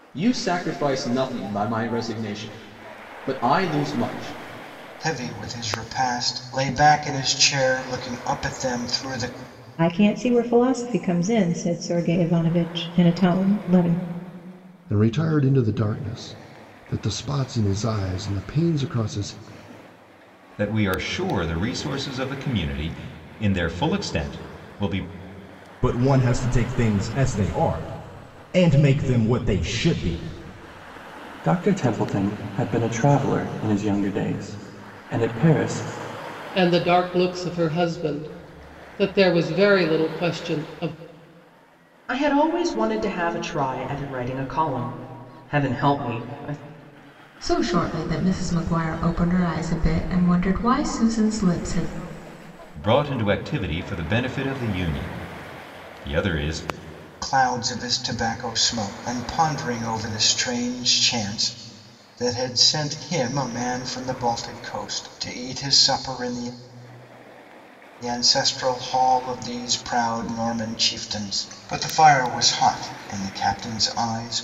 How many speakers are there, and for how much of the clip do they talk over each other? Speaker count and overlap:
ten, no overlap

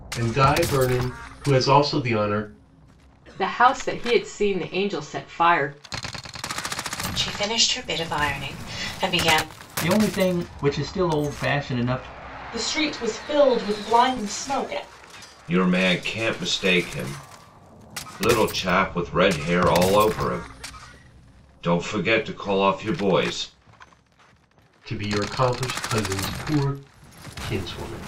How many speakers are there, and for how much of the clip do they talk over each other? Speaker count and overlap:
six, no overlap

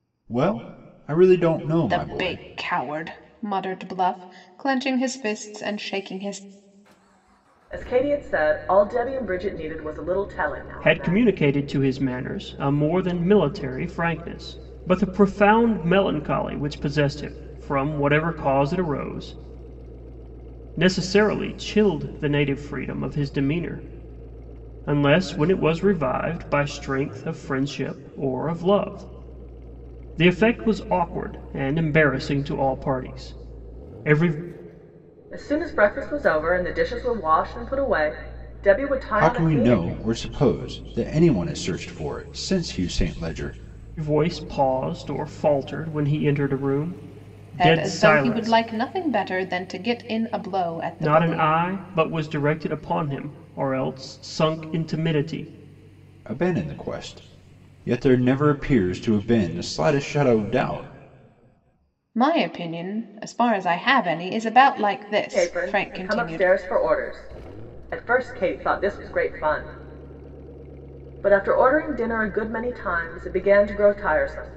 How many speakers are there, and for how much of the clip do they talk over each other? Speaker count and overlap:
four, about 6%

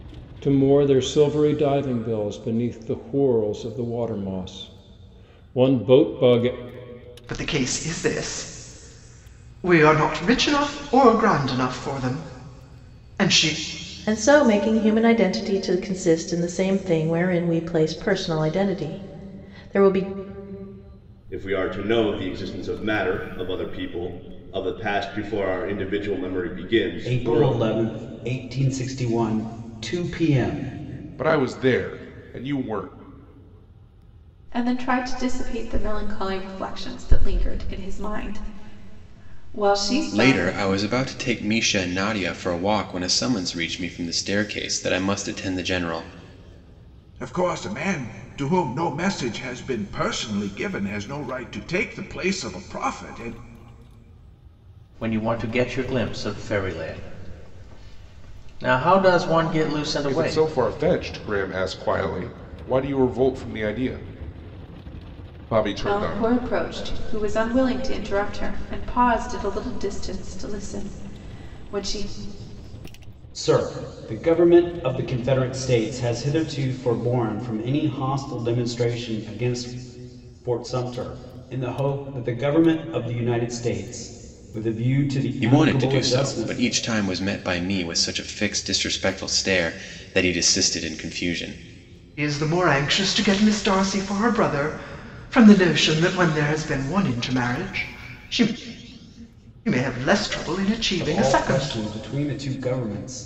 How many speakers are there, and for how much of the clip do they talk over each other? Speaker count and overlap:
ten, about 4%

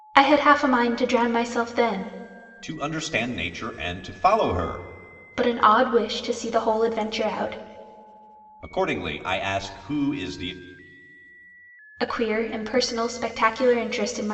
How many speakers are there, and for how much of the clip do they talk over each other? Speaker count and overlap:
two, no overlap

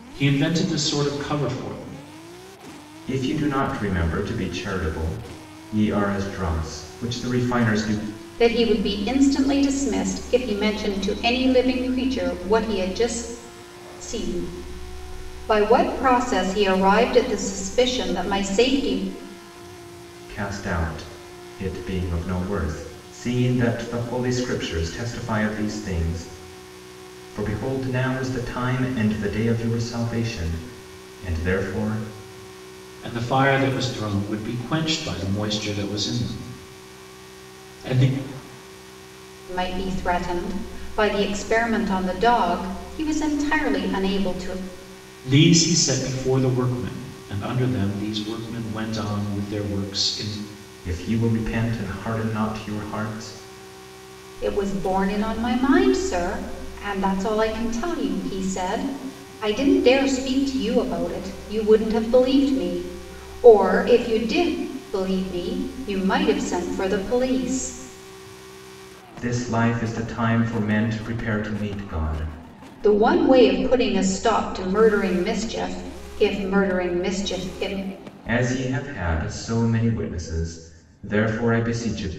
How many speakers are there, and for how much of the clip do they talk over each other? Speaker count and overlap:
three, no overlap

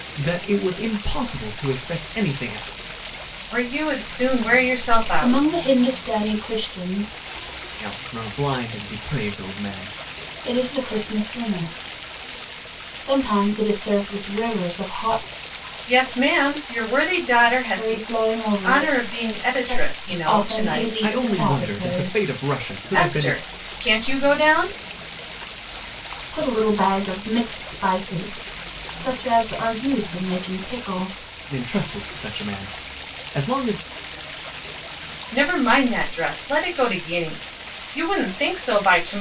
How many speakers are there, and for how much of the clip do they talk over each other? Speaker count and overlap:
three, about 11%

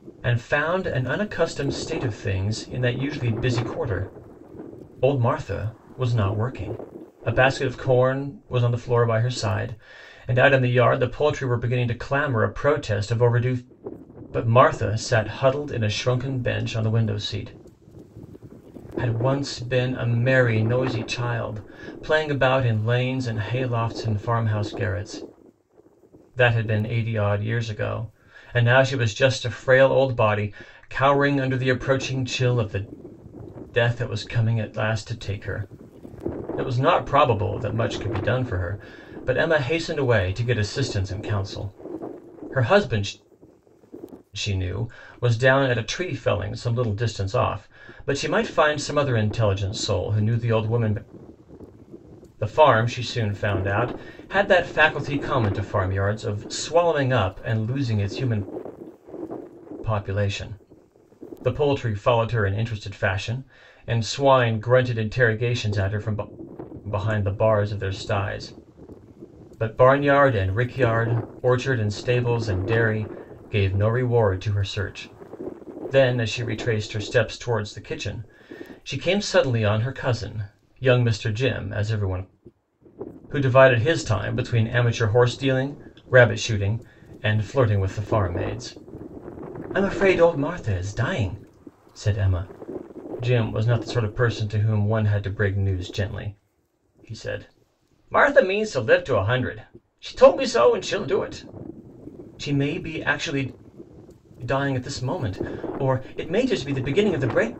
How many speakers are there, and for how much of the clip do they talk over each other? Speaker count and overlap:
one, no overlap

